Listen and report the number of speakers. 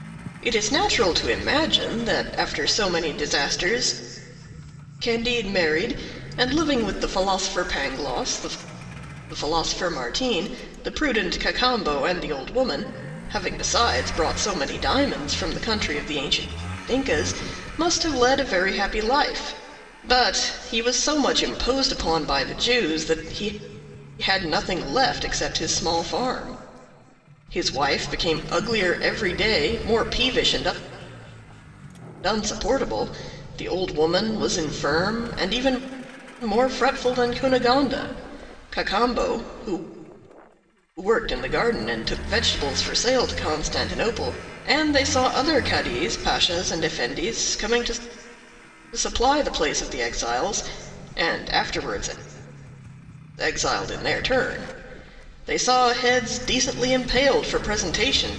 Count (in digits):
1